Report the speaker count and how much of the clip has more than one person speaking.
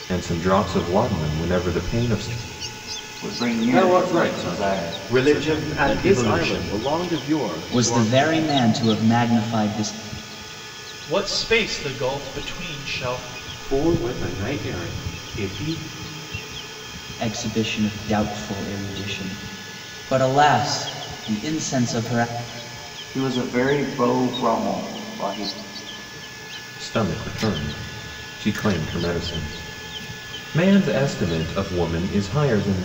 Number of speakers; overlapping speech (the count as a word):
seven, about 11%